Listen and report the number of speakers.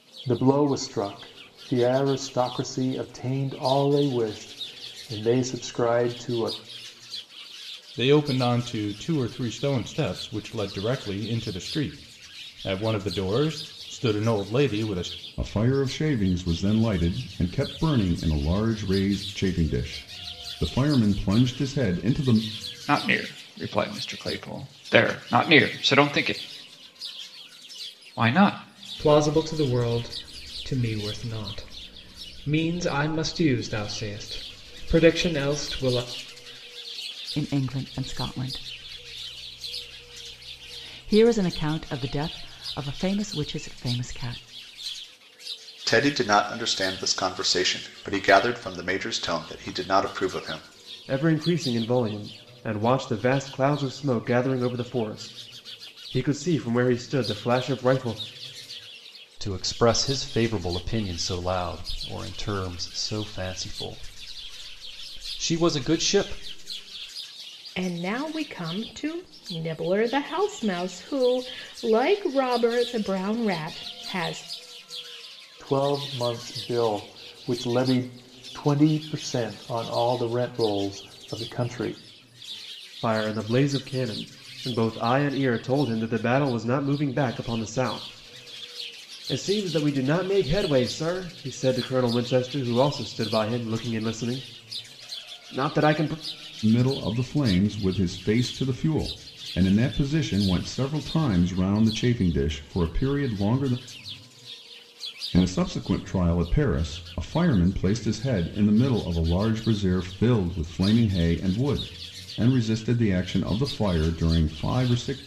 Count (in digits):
10